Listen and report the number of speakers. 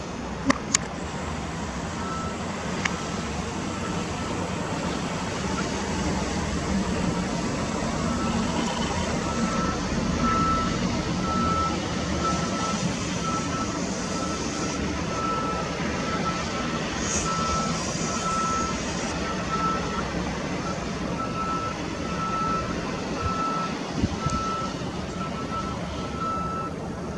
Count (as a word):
zero